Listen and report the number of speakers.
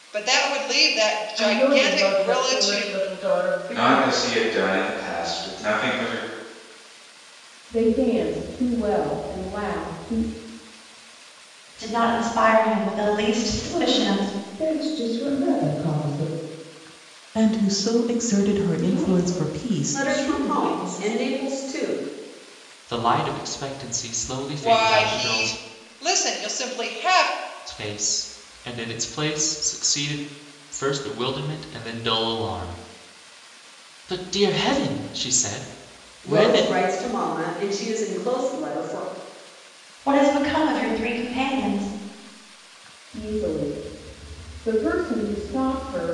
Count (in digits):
10